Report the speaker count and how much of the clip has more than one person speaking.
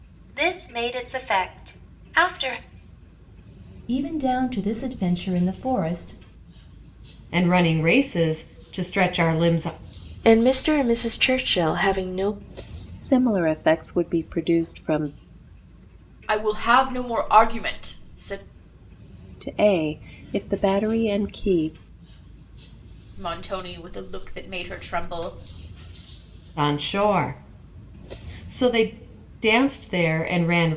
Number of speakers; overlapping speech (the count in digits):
6, no overlap